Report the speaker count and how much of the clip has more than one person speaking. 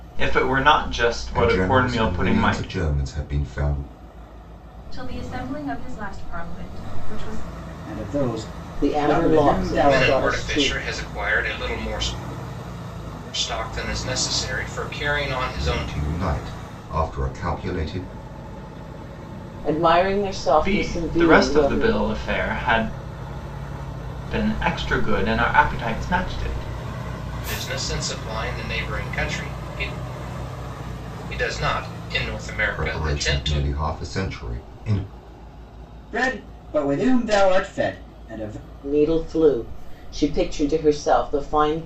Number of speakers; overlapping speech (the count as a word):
six, about 15%